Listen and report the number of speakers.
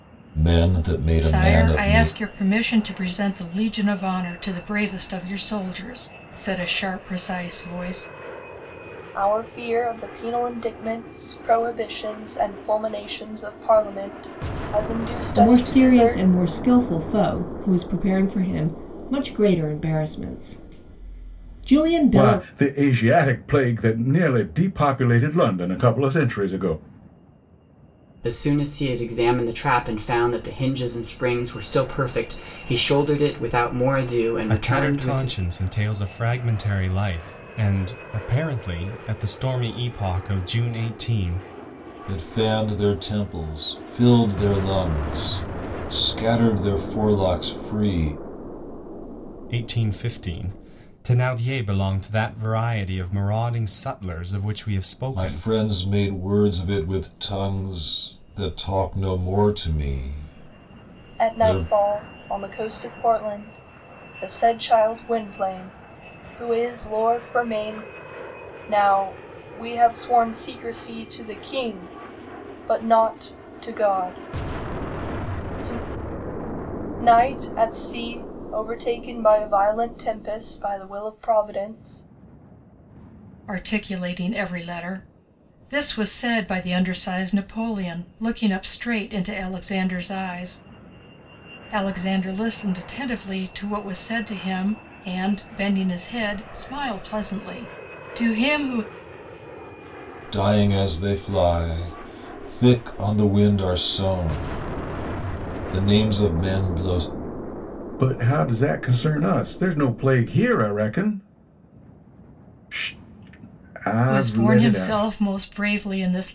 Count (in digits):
7